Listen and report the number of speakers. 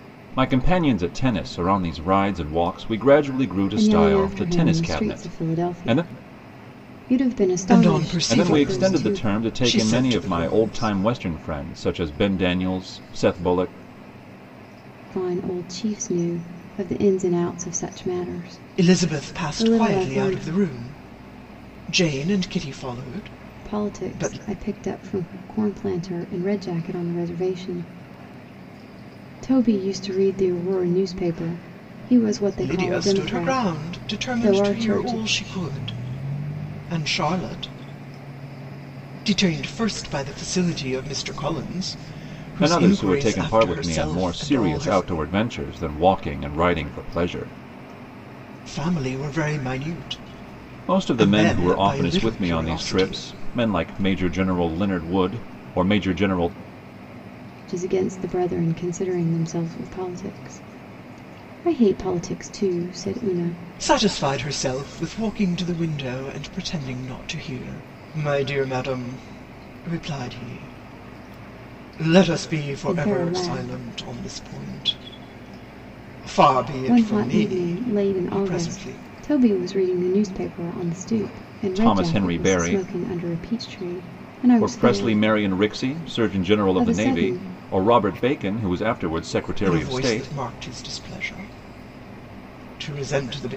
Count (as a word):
three